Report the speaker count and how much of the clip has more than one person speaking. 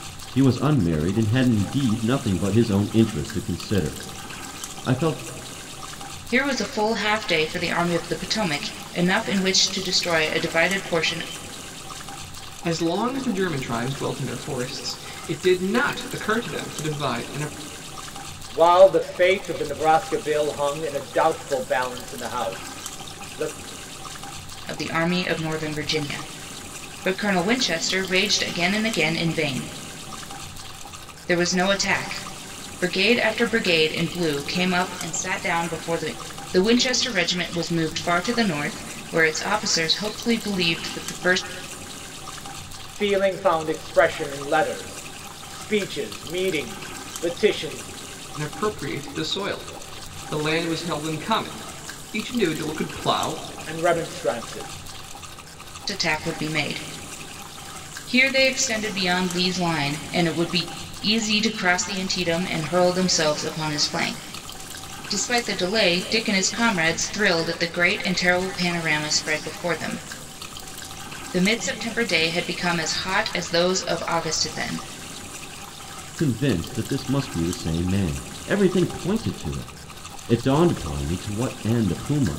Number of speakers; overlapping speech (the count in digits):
4, no overlap